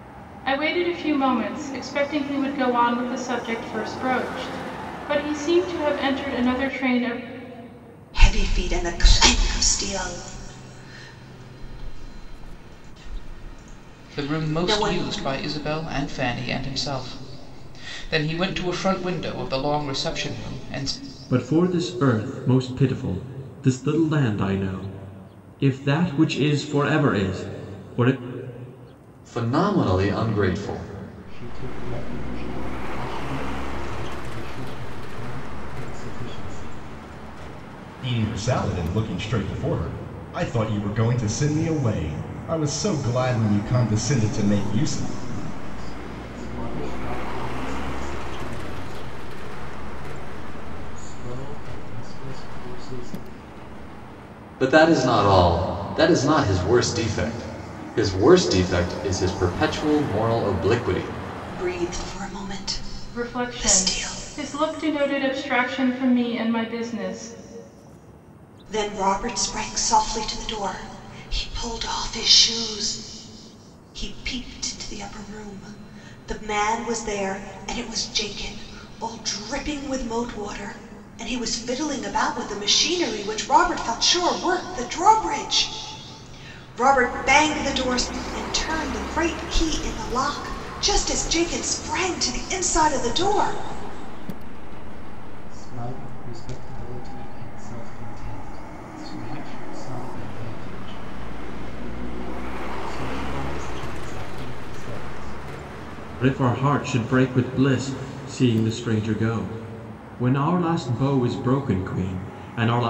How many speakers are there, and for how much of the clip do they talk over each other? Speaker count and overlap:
7, about 3%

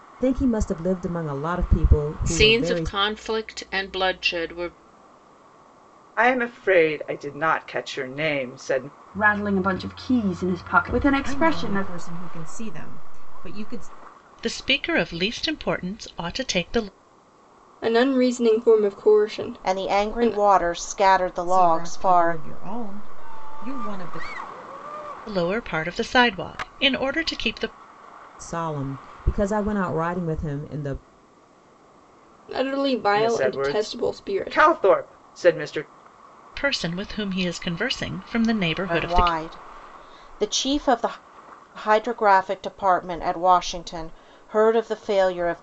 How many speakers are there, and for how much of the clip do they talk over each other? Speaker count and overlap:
8, about 11%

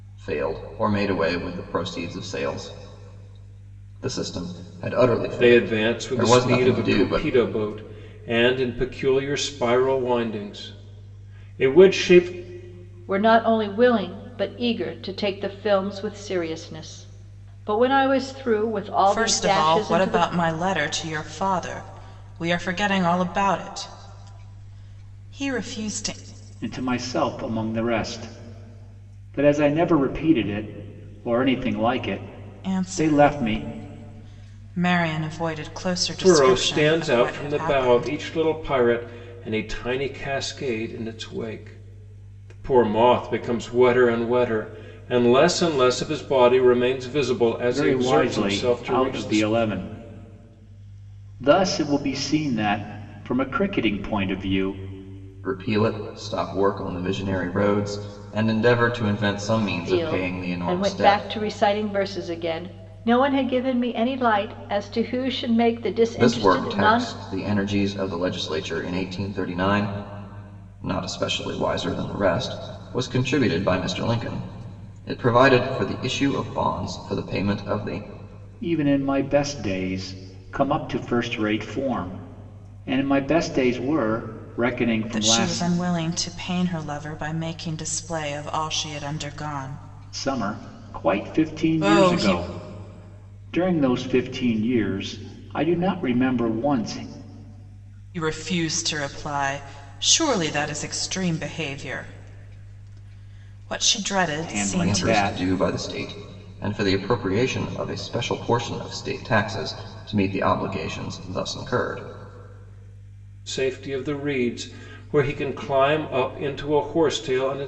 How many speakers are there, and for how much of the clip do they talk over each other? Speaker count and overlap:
5, about 12%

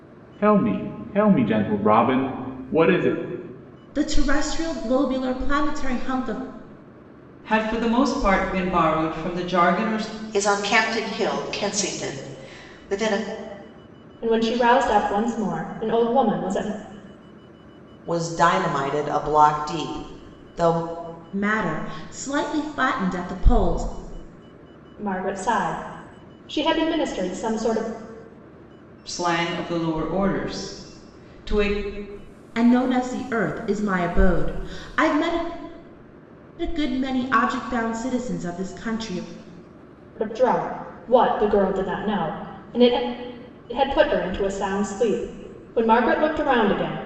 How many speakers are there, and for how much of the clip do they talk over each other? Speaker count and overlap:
6, no overlap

